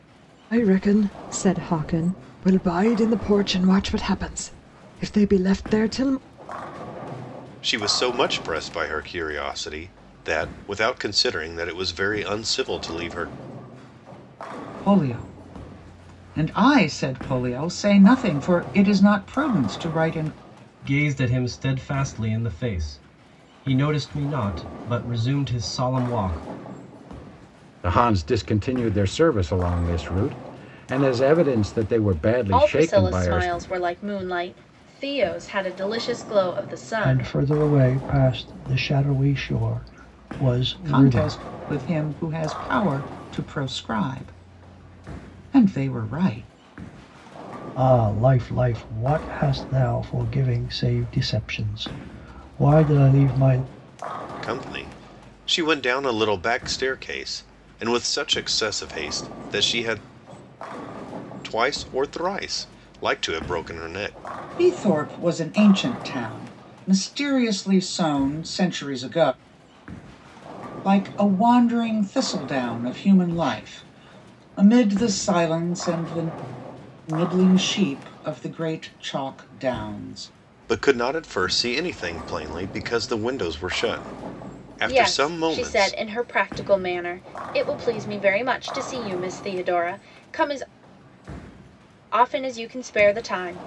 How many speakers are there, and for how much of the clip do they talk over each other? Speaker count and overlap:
7, about 3%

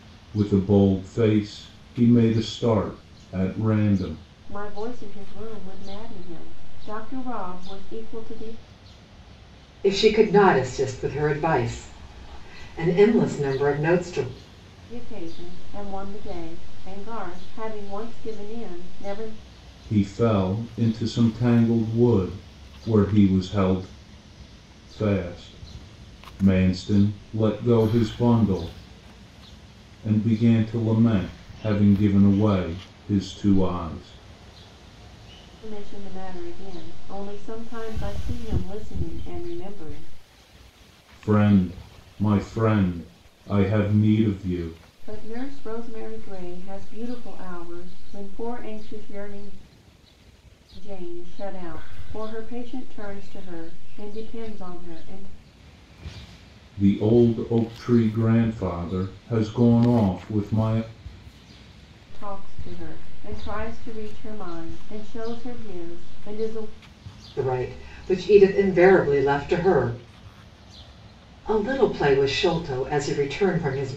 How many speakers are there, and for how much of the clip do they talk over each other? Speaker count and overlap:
3, no overlap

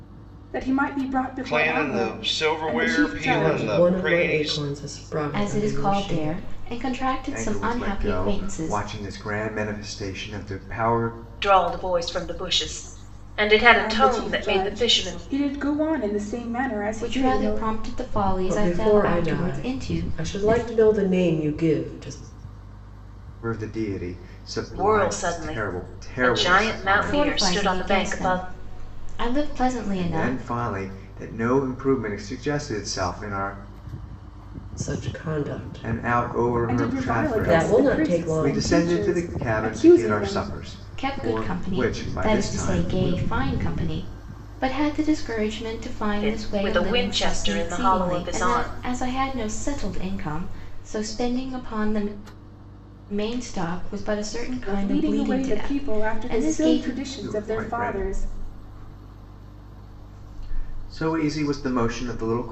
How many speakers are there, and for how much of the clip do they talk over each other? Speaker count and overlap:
6, about 44%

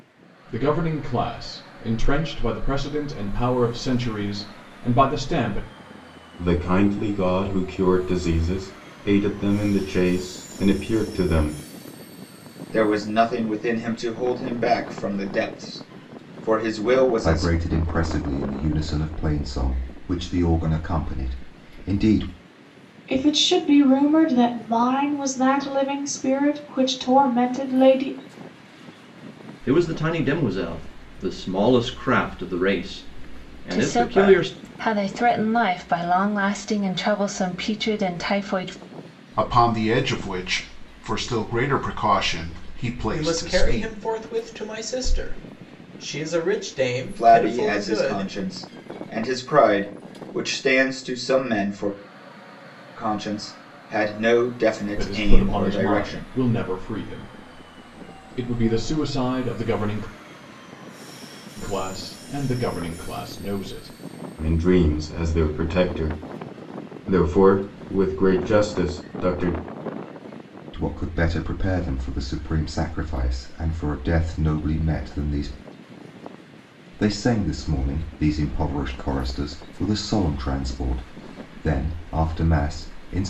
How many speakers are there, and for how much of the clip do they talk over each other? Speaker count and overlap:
9, about 6%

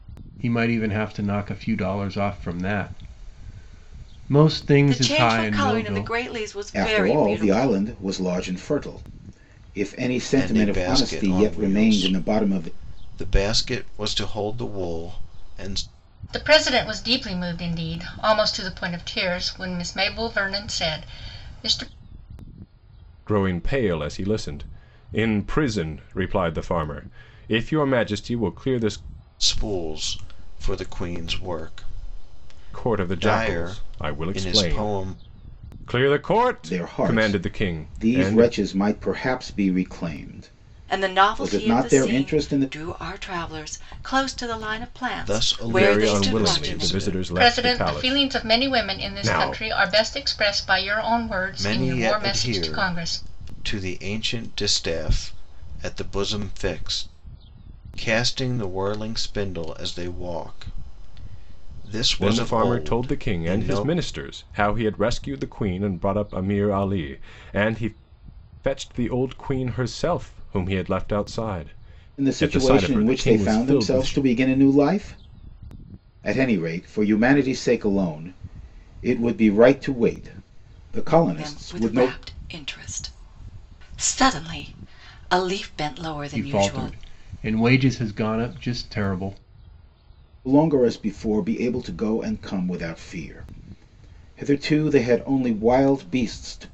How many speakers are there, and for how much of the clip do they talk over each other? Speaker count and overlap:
6, about 23%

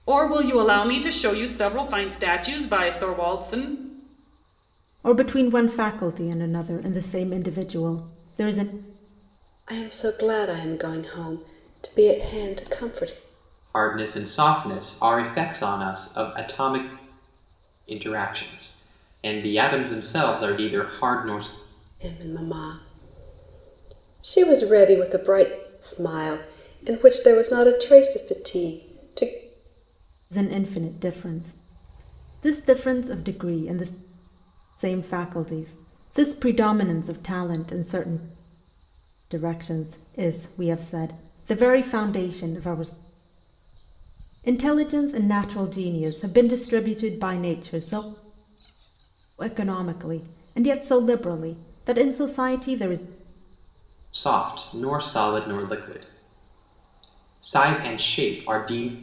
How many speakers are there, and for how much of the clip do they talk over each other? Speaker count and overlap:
4, no overlap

